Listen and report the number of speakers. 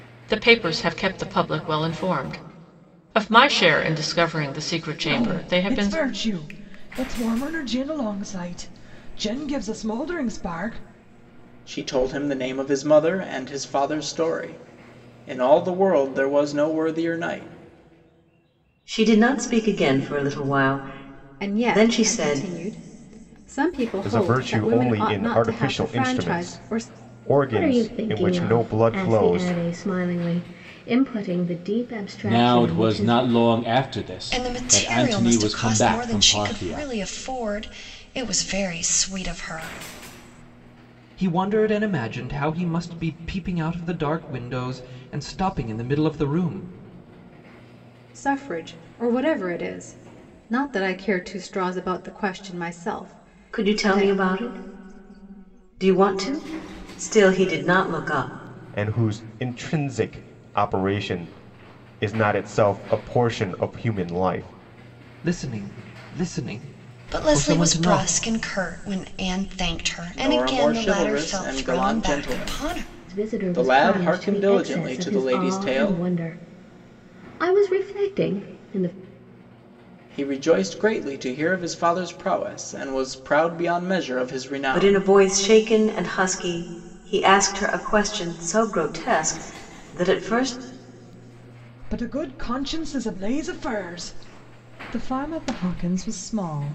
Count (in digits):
10